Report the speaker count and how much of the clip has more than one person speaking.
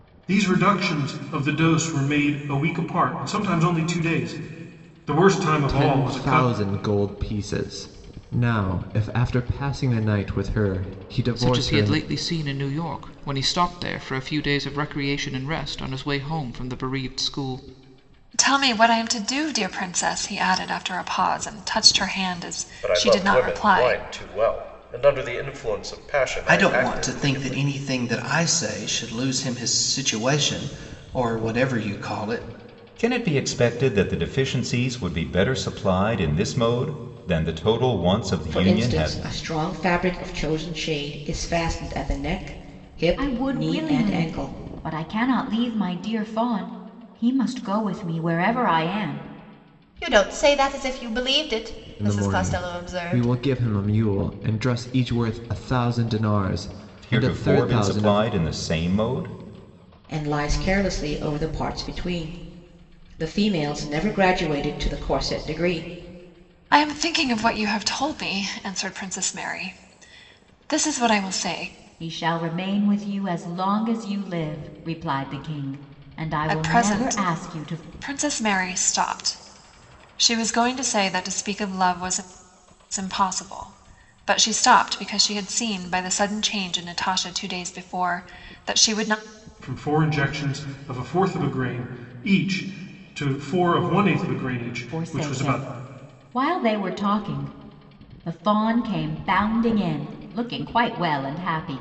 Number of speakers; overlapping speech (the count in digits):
10, about 11%